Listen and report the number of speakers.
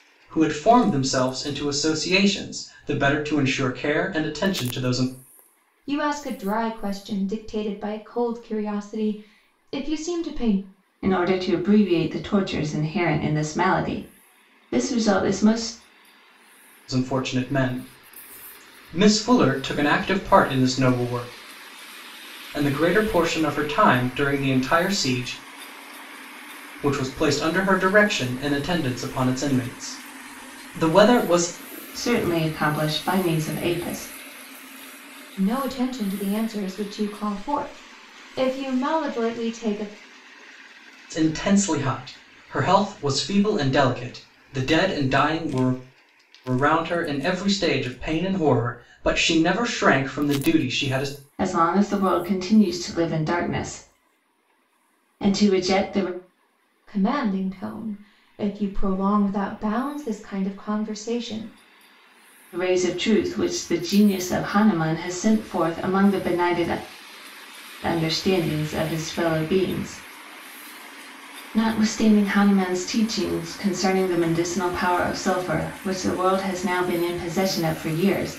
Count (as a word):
three